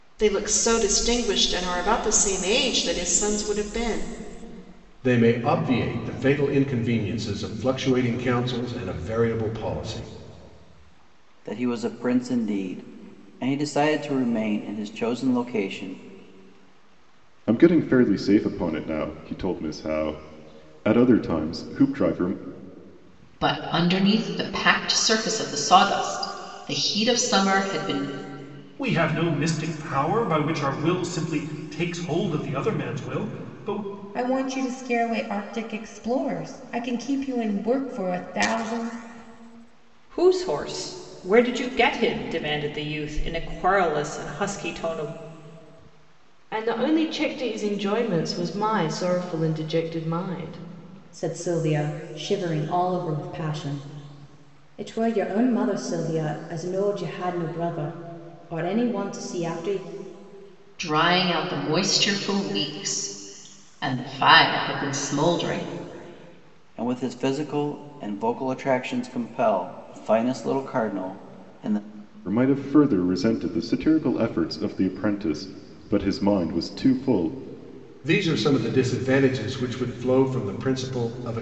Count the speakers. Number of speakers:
ten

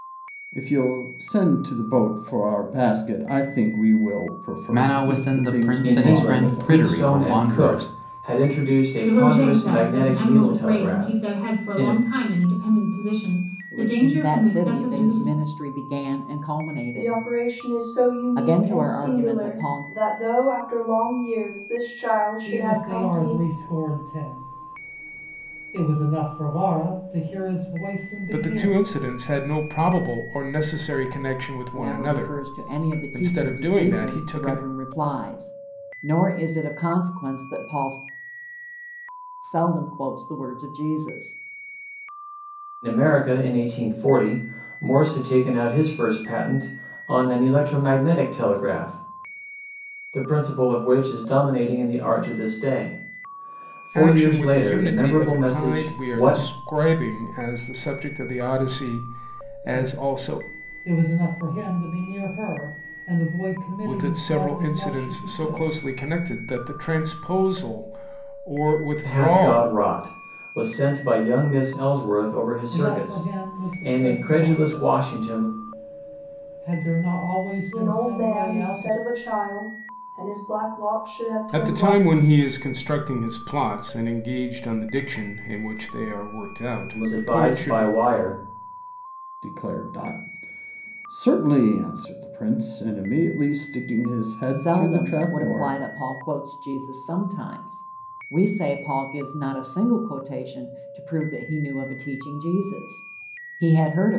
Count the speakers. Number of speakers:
eight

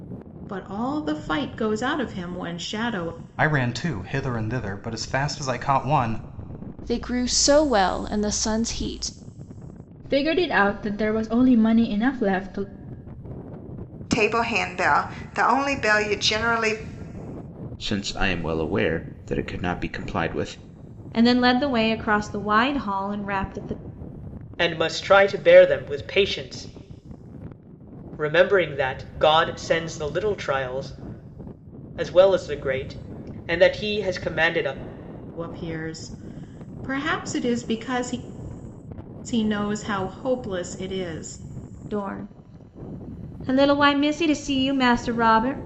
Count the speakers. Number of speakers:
eight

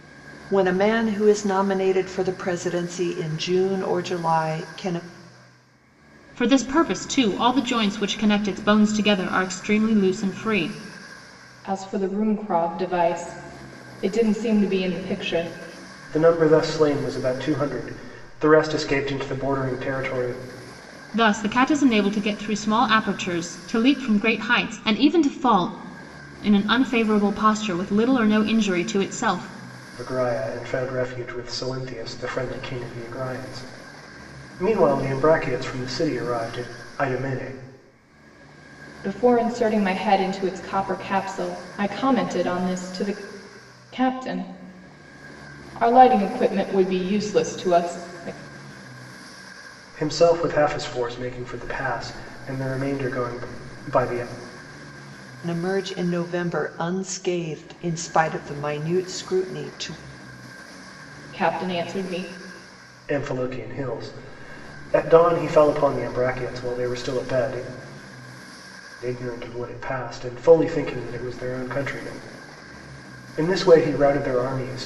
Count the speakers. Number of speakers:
four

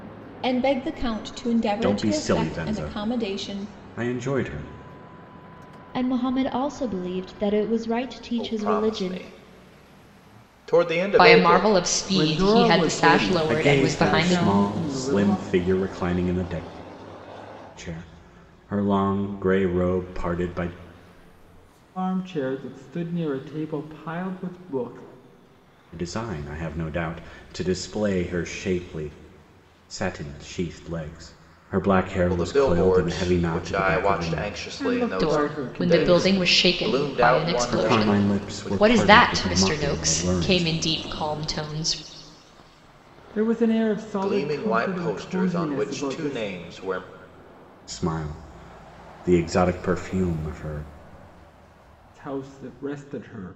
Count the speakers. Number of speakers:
six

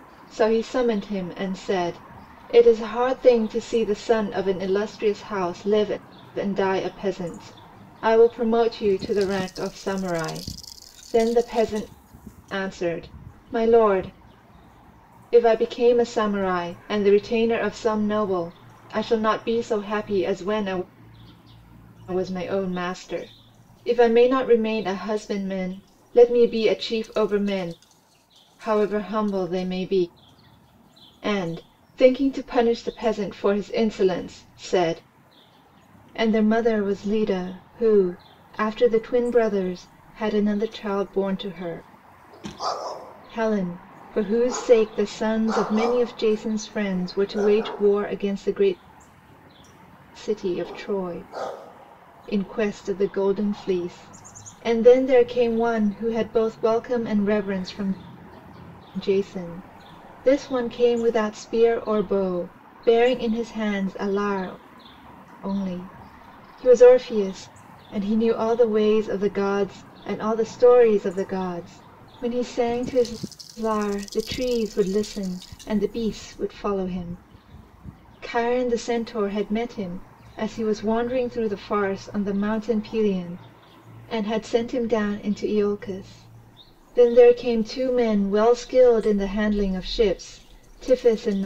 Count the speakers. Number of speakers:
one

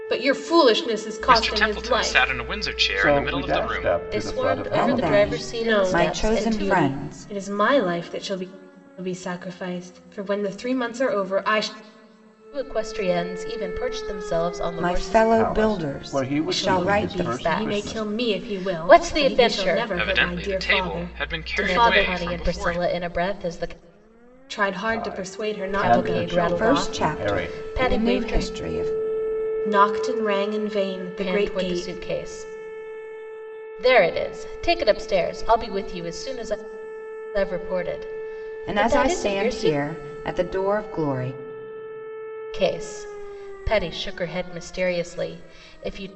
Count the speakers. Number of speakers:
five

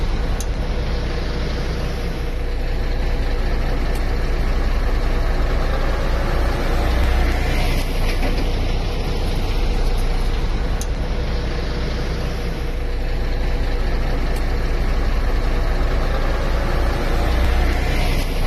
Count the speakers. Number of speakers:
zero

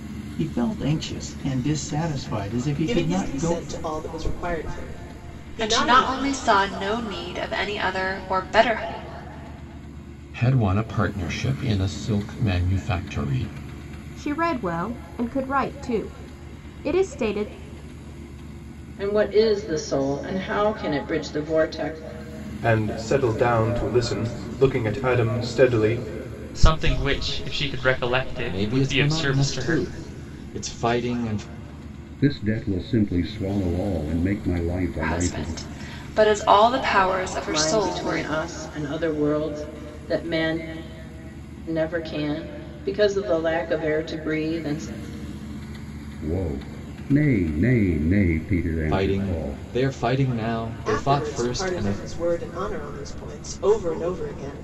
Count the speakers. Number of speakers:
ten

